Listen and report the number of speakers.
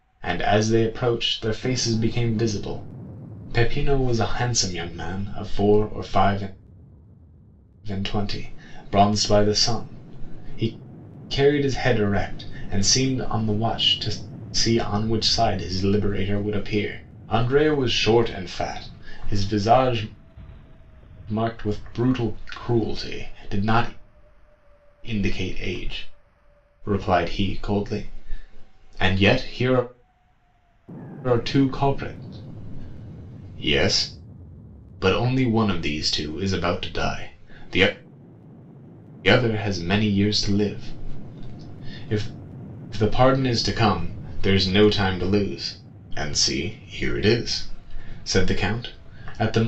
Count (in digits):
1